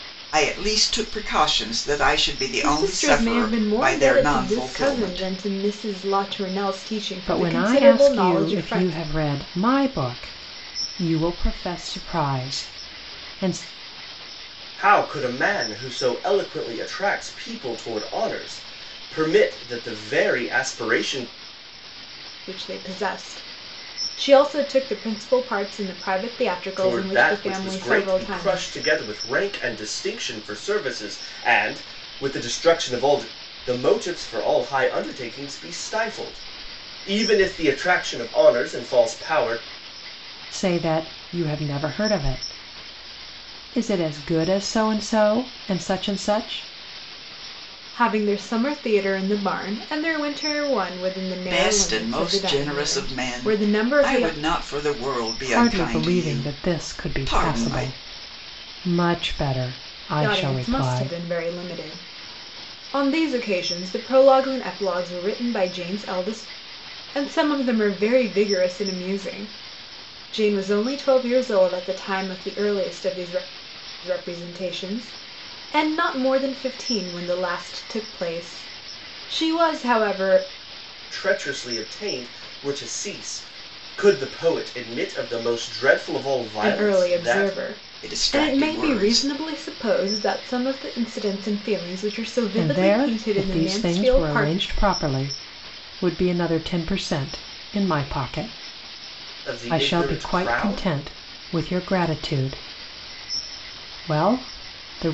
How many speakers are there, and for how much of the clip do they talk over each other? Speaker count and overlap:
four, about 17%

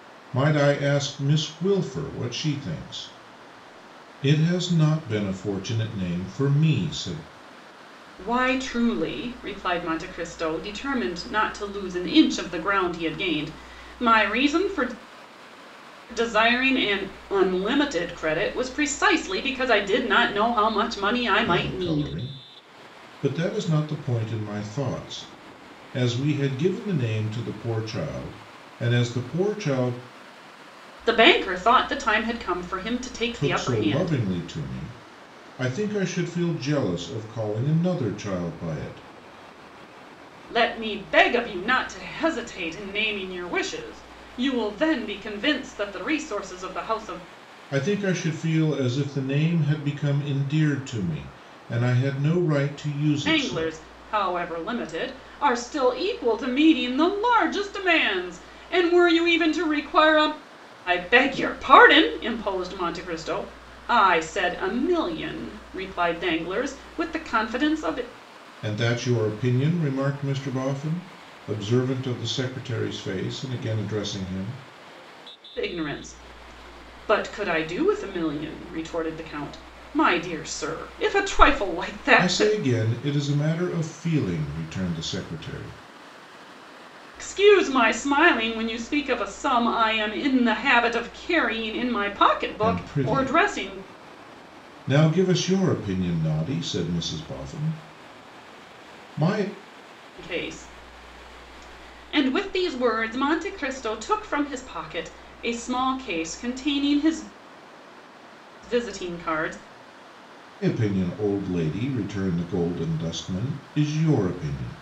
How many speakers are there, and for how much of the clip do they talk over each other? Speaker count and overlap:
two, about 3%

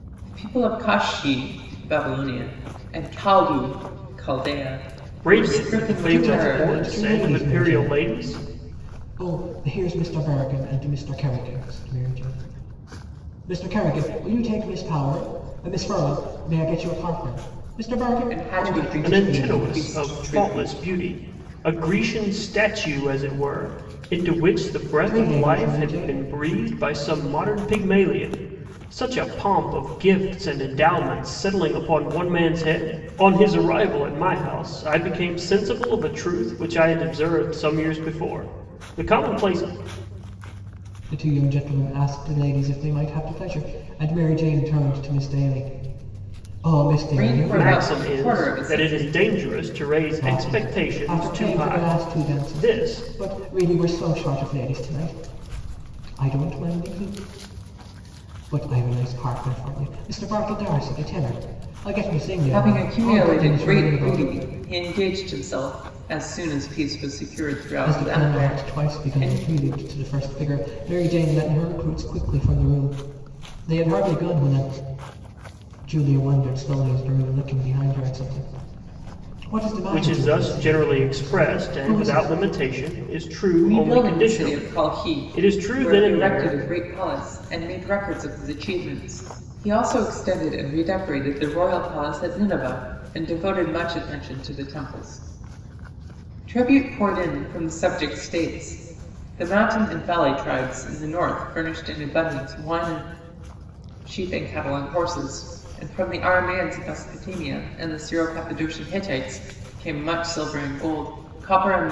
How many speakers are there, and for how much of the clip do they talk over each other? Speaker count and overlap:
three, about 19%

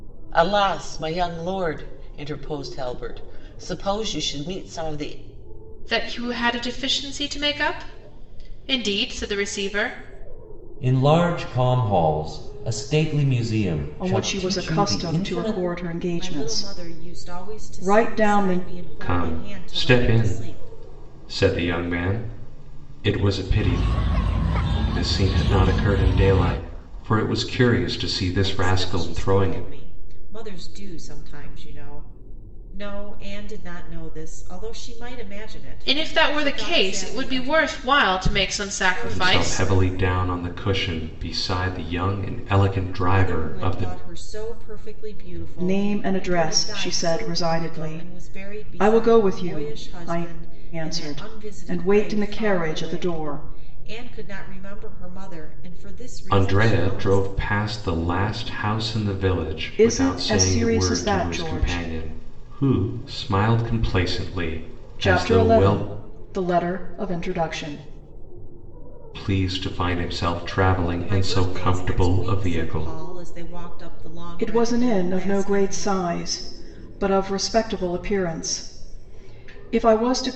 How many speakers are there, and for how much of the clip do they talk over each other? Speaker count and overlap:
six, about 32%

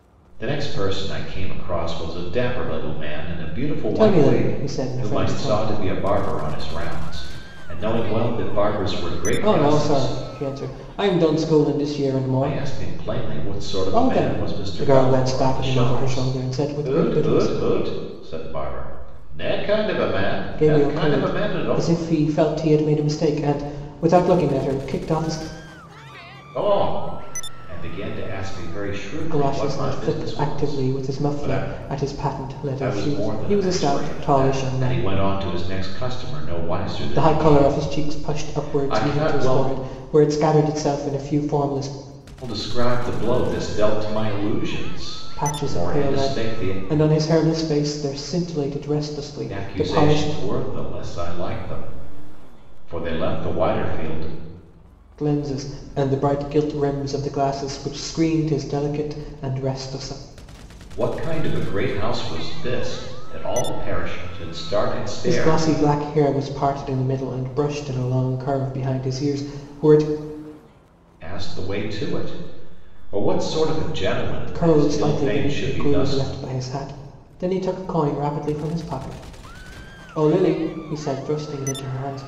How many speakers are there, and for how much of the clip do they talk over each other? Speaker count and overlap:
two, about 24%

